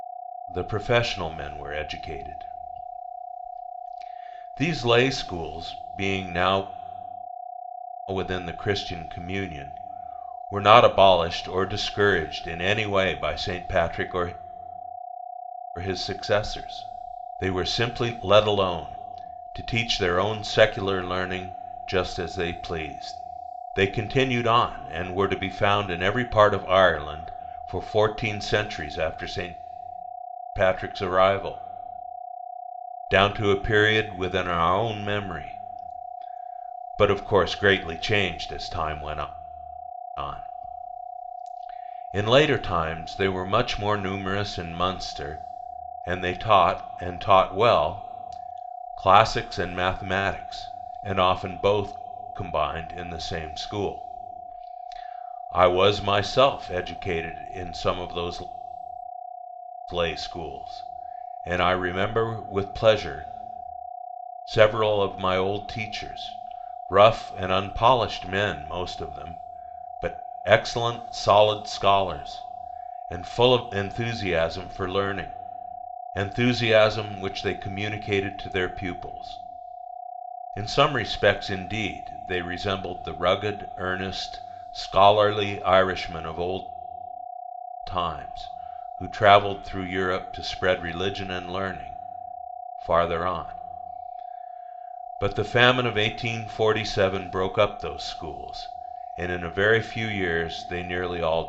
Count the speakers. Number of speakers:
1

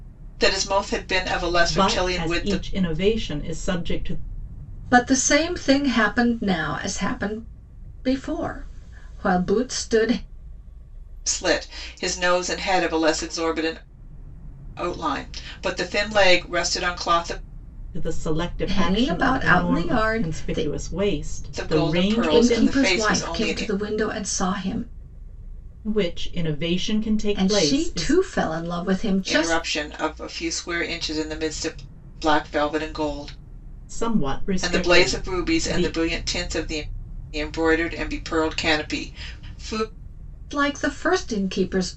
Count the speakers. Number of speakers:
3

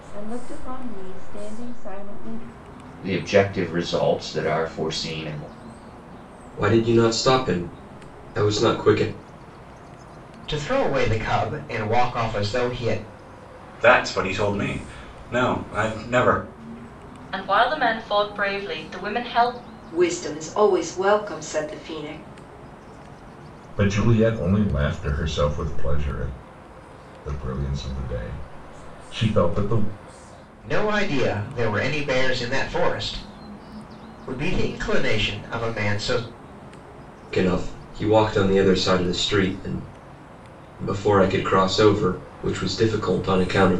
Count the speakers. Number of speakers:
8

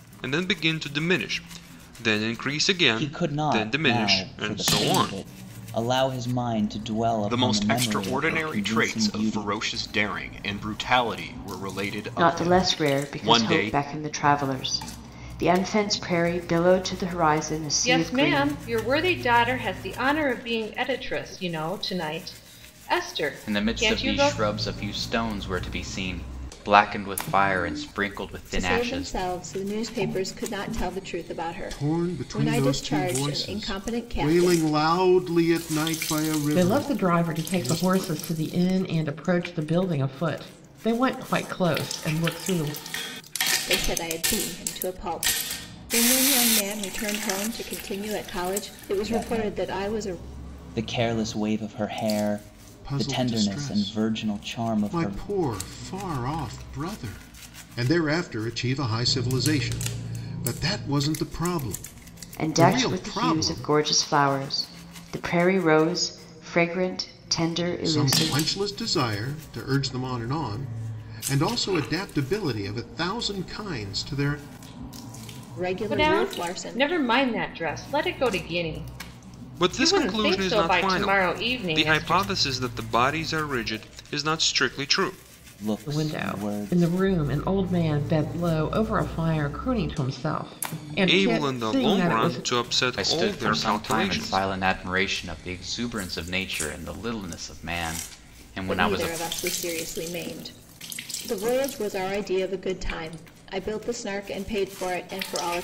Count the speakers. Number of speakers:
9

